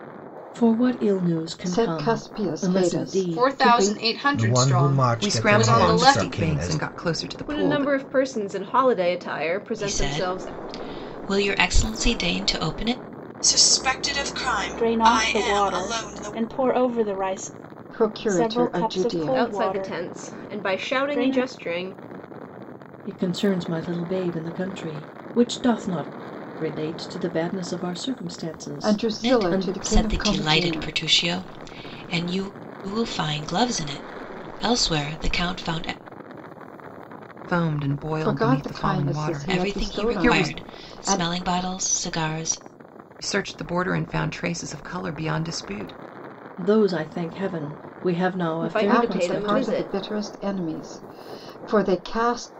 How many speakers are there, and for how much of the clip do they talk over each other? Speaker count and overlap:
9, about 34%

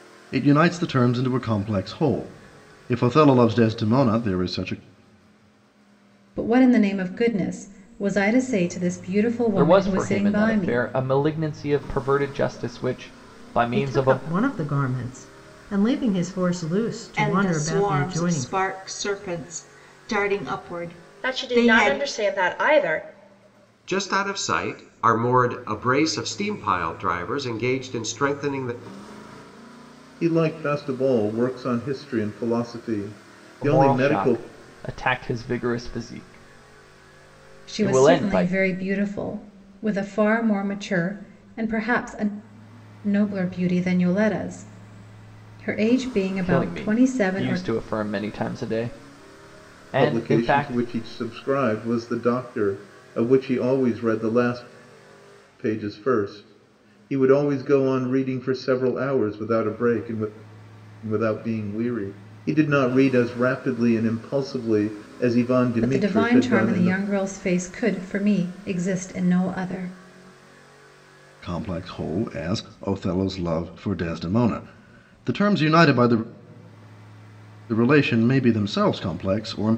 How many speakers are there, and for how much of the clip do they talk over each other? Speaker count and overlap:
8, about 12%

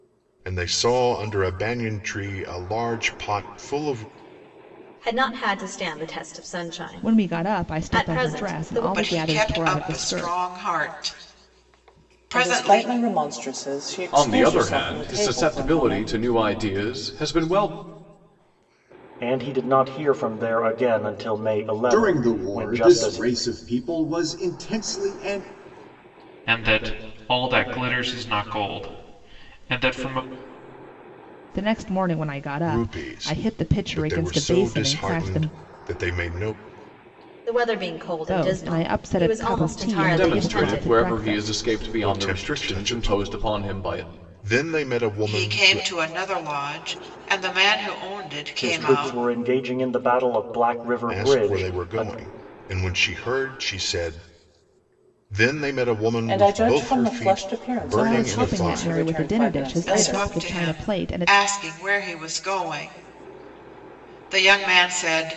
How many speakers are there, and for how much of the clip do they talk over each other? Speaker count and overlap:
9, about 36%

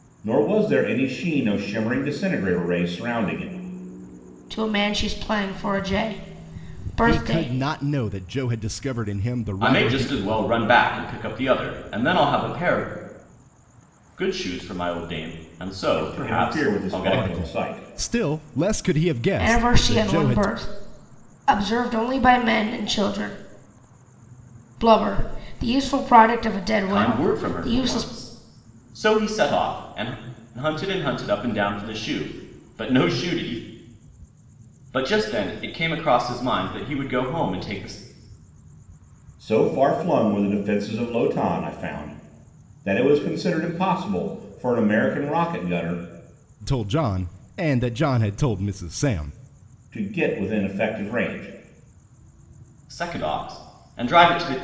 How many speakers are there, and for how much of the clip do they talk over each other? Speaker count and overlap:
4, about 10%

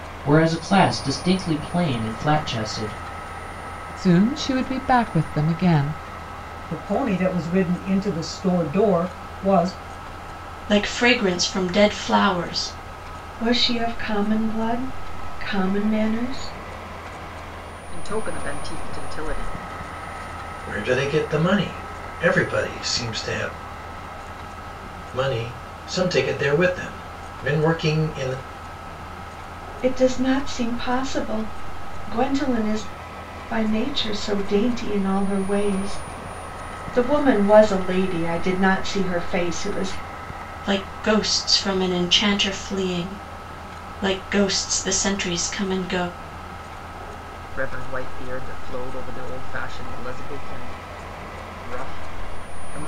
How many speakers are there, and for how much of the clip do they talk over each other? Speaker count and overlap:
7, no overlap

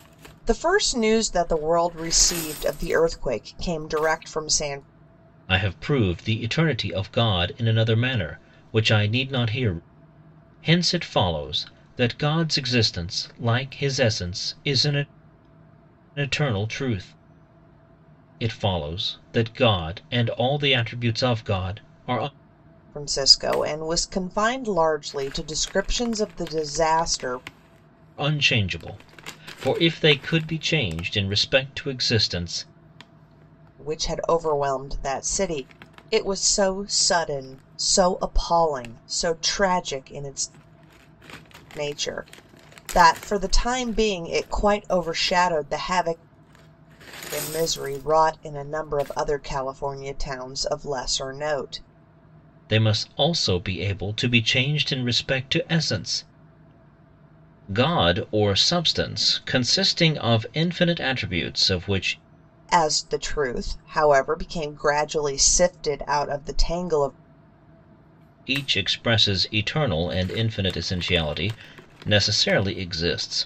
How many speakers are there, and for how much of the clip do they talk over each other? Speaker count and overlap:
2, no overlap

